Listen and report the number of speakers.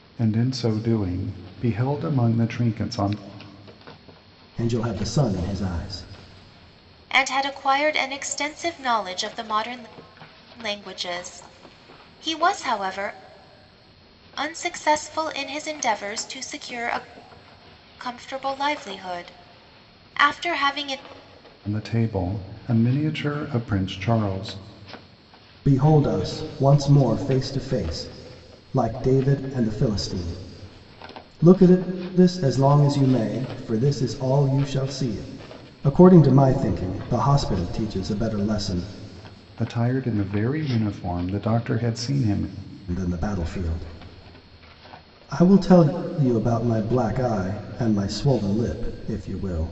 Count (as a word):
three